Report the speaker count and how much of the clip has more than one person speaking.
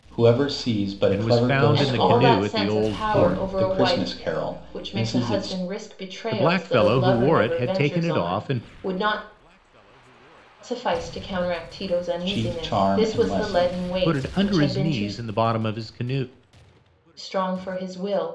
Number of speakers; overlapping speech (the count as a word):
three, about 51%